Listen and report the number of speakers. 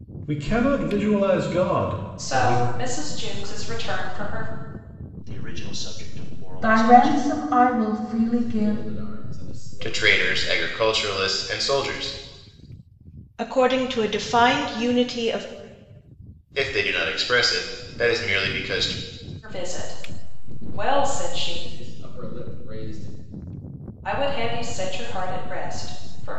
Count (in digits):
7